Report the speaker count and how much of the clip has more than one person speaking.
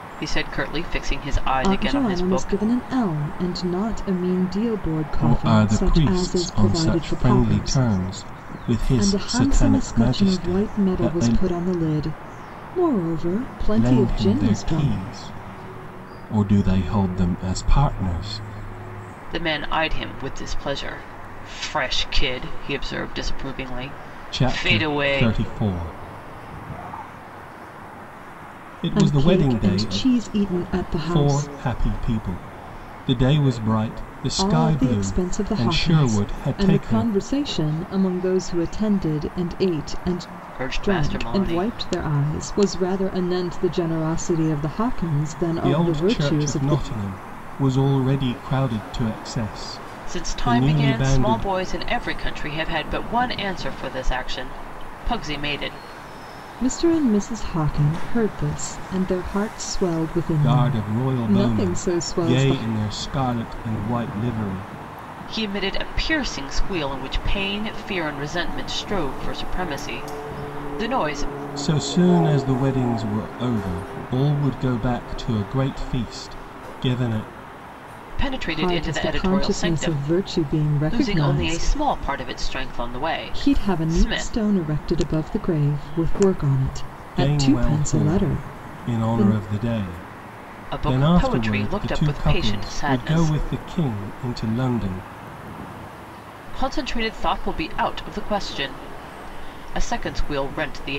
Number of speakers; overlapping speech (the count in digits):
3, about 27%